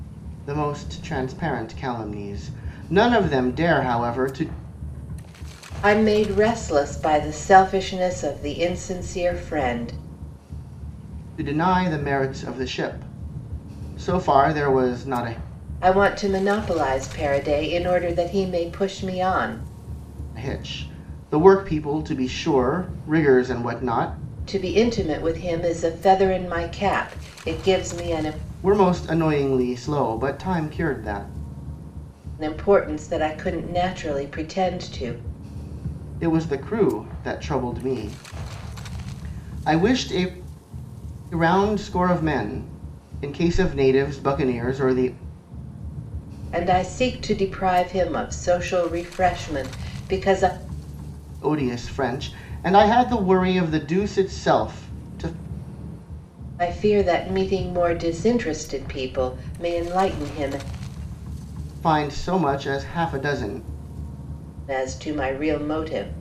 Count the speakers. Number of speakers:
2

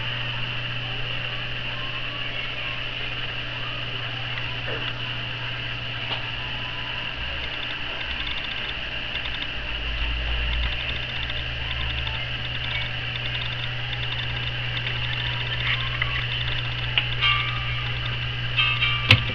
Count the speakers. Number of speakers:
0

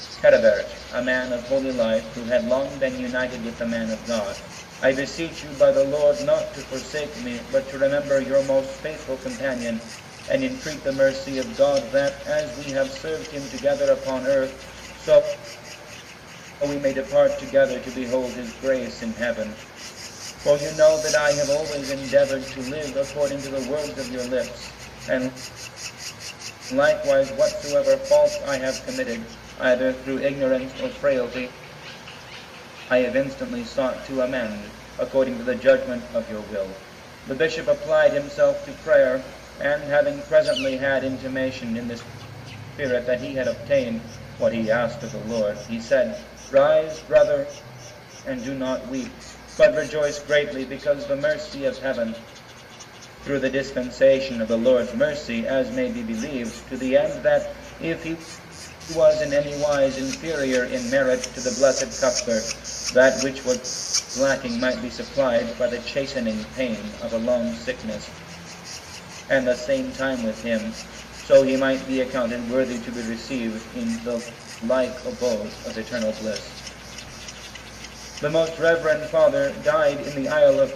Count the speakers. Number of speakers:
1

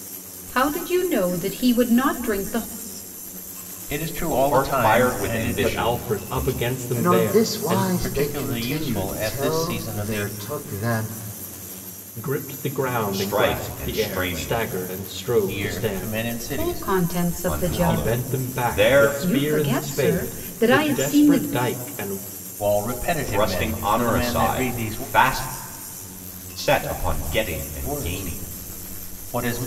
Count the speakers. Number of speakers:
5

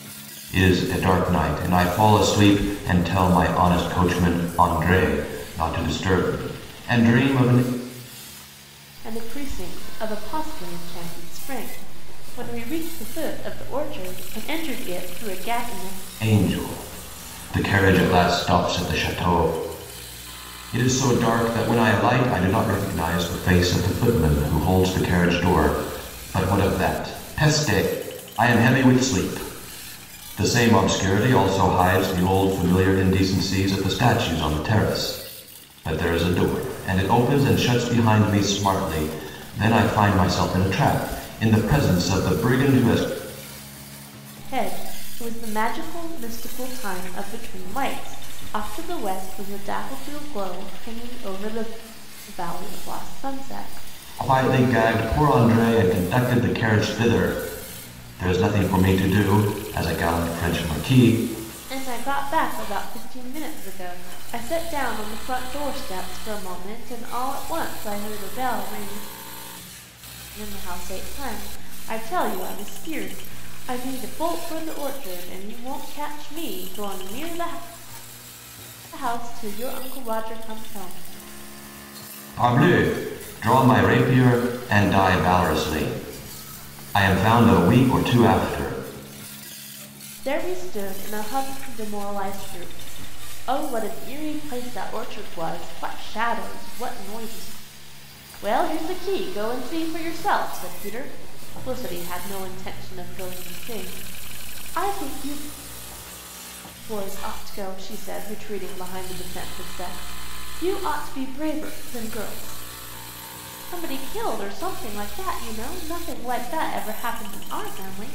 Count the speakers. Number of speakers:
2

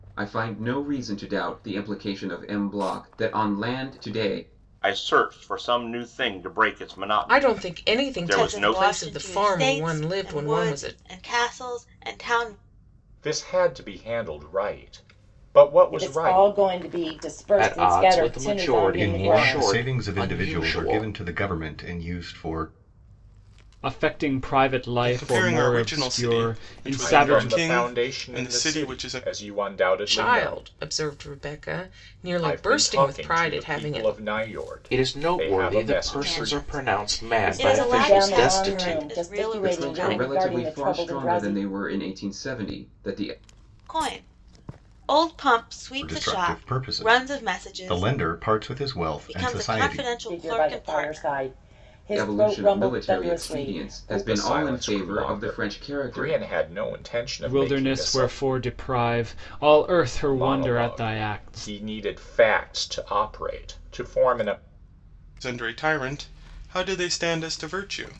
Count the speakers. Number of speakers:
10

